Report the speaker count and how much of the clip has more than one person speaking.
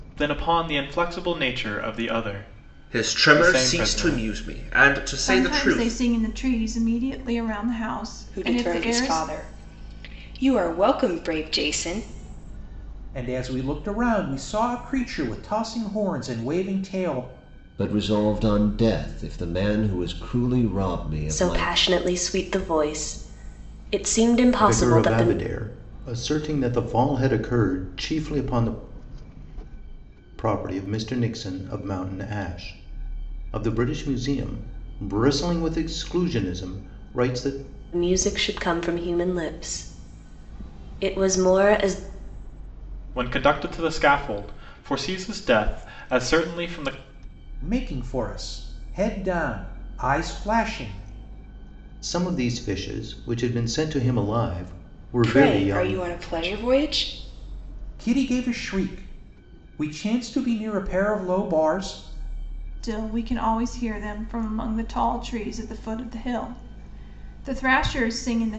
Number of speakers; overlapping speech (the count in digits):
8, about 8%